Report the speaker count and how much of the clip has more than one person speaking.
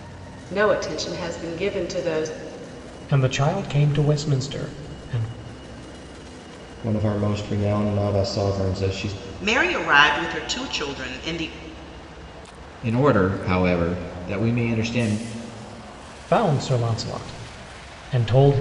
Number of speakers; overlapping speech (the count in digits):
5, no overlap